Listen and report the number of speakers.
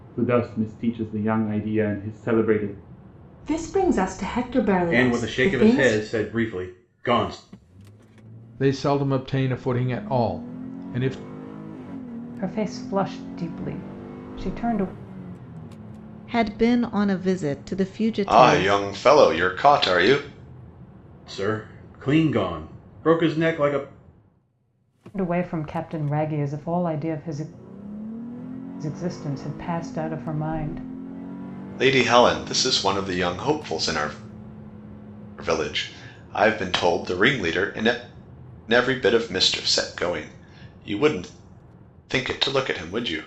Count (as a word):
seven